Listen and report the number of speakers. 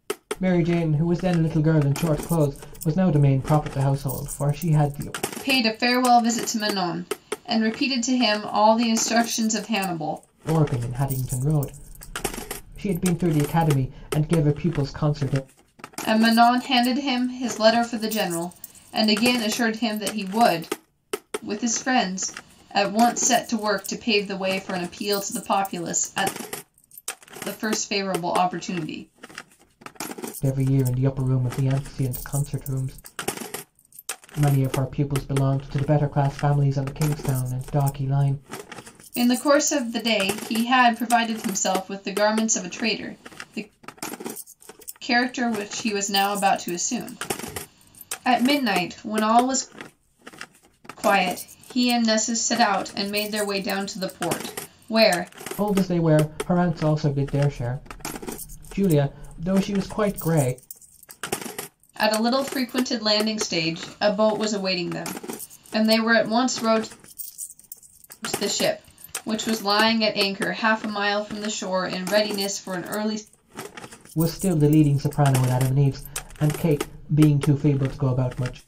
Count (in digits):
2